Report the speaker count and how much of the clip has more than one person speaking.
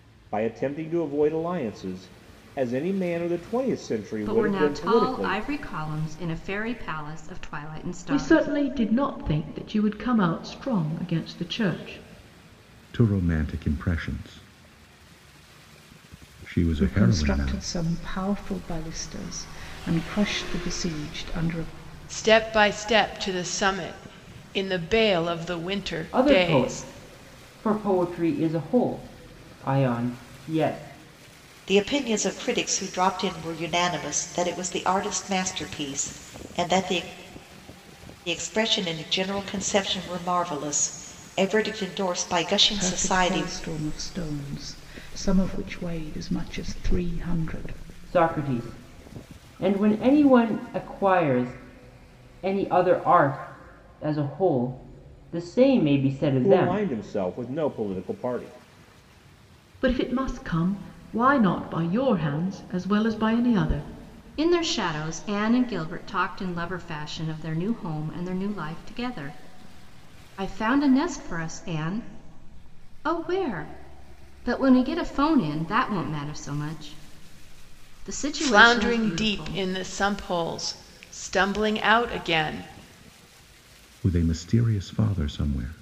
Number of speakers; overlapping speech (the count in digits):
8, about 7%